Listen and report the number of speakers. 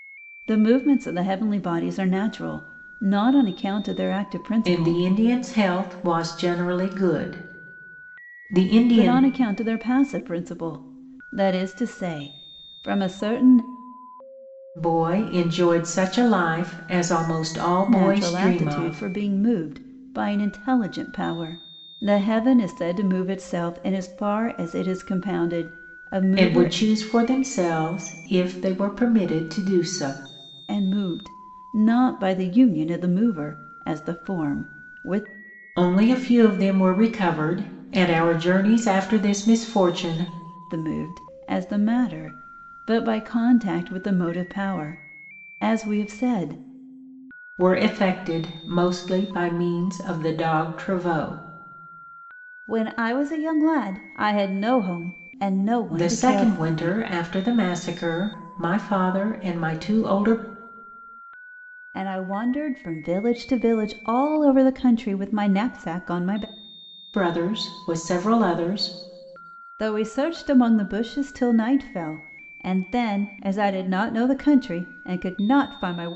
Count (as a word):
two